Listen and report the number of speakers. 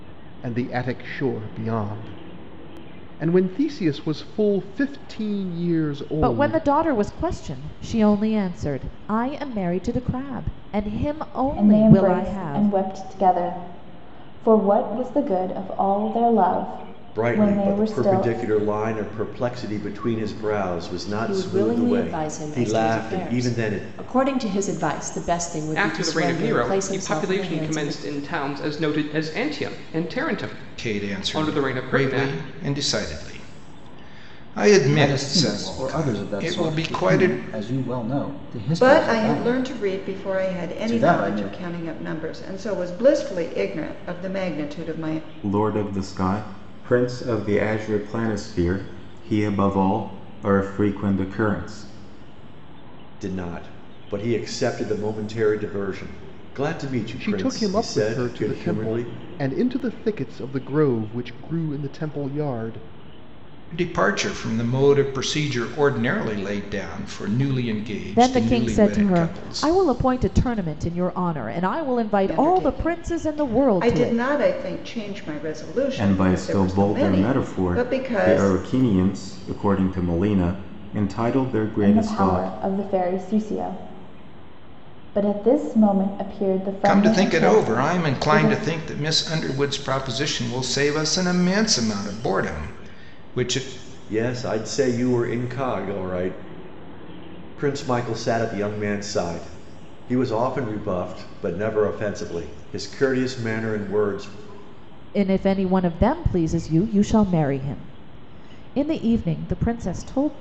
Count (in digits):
10